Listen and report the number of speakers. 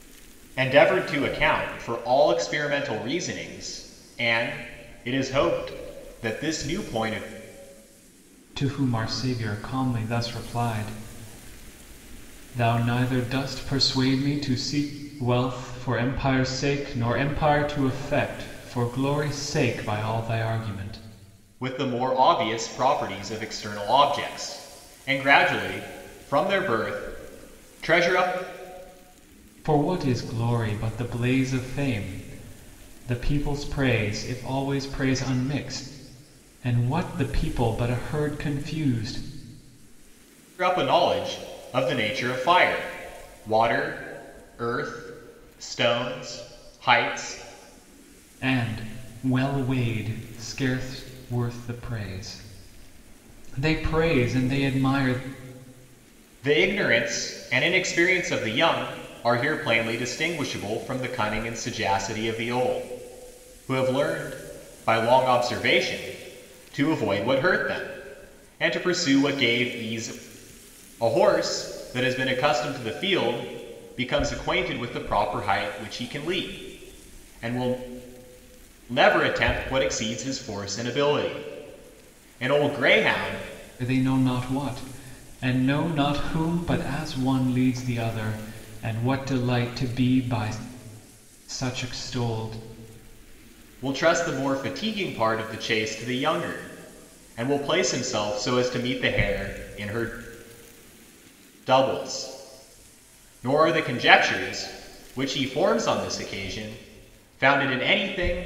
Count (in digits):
2